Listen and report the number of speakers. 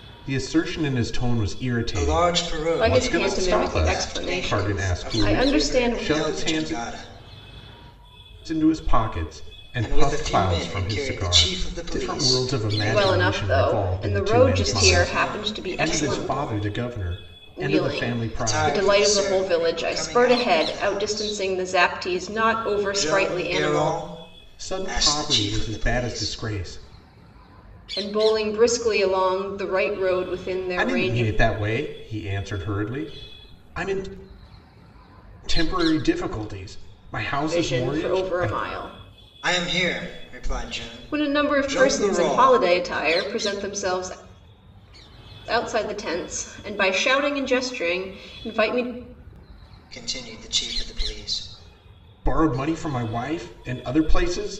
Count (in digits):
3